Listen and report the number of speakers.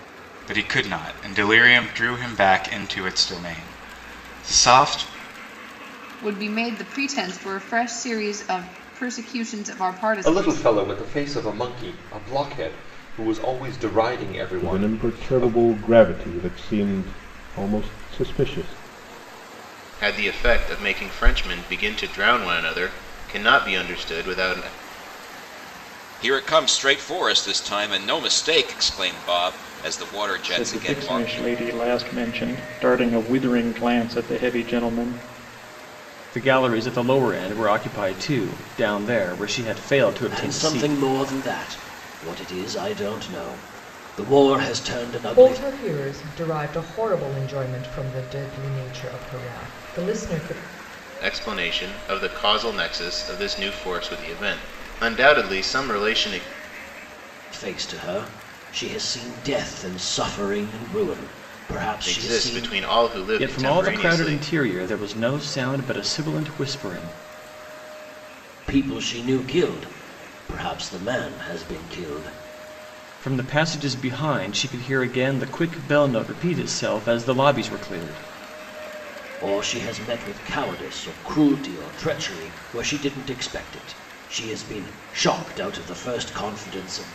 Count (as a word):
ten